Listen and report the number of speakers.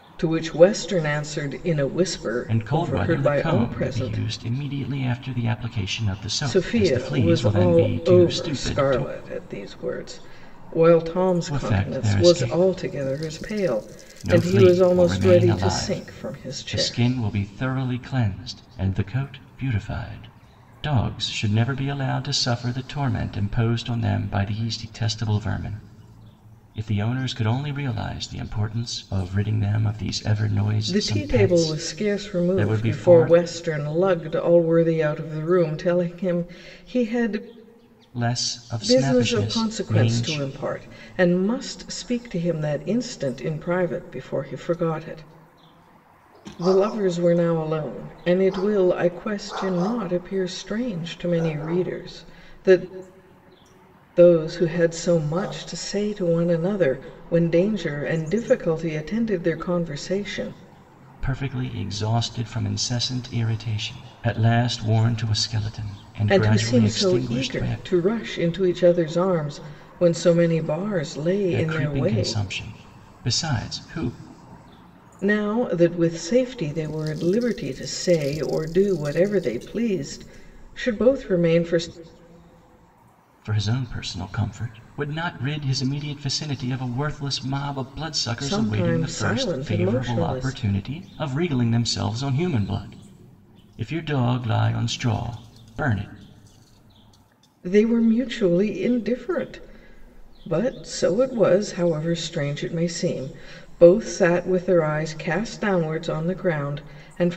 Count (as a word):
two